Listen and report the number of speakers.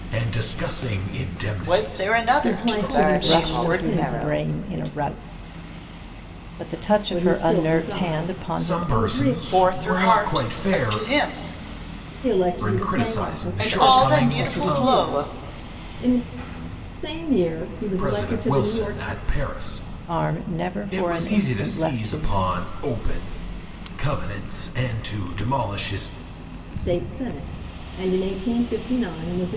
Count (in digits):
5